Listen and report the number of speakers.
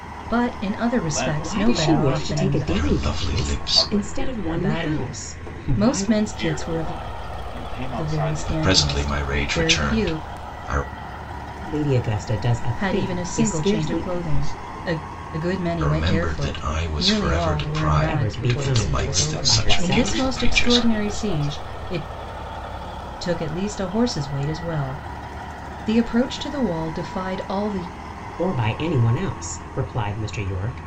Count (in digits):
4